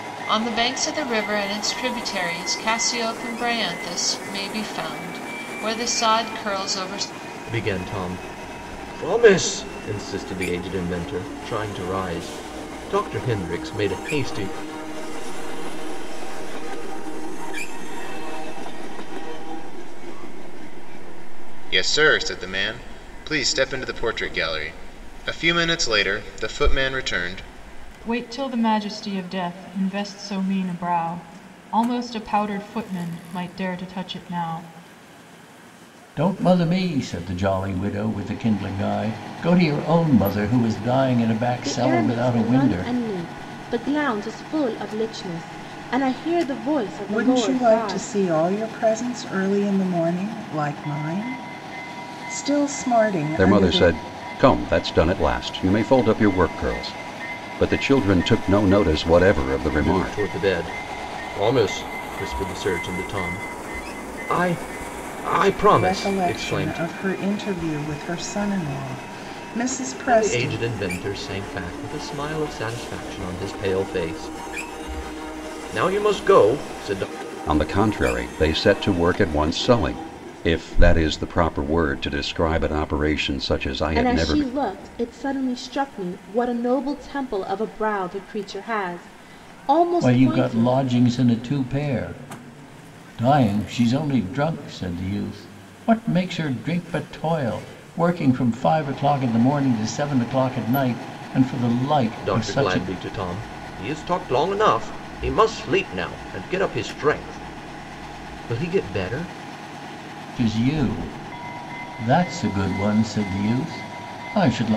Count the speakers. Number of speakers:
9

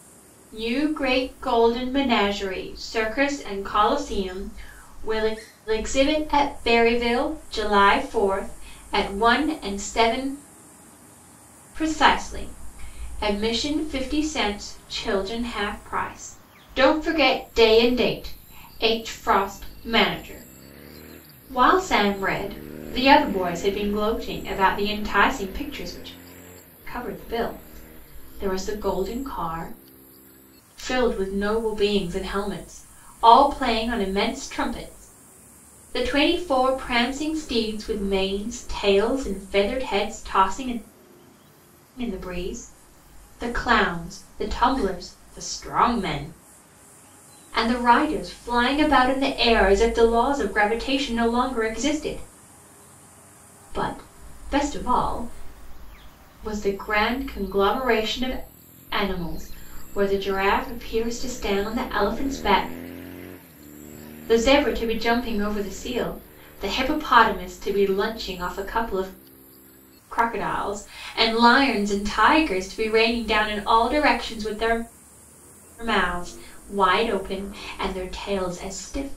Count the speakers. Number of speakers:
1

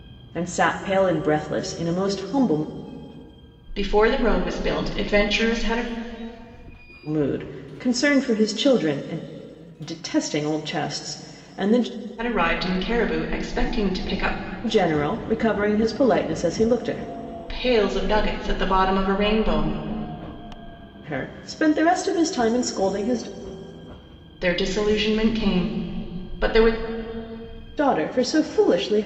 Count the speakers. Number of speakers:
2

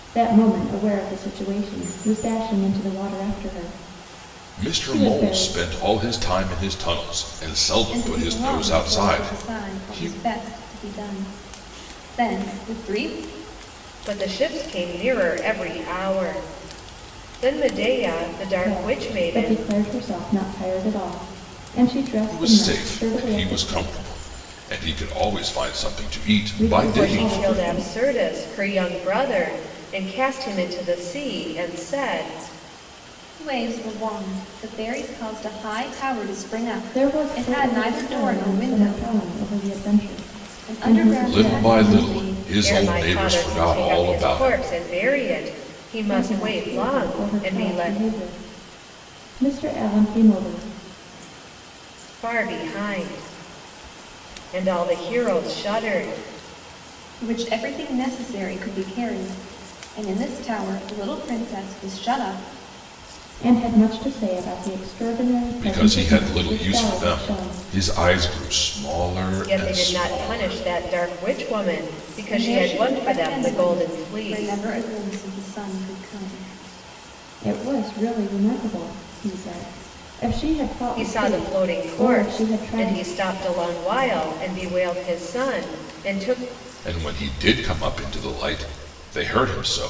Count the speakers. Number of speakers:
4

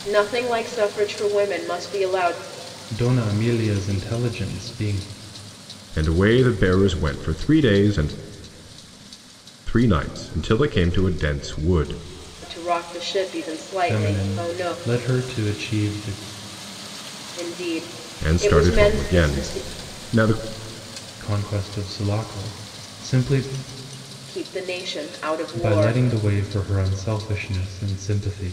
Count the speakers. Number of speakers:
3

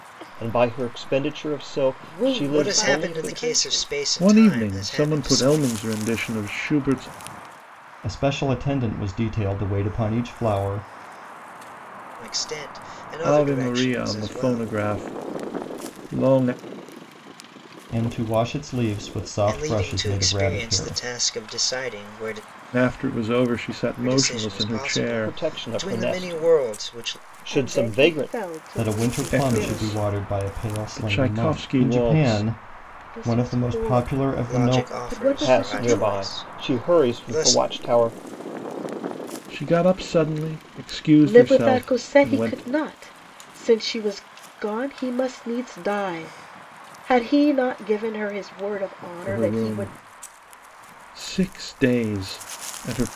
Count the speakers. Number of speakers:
5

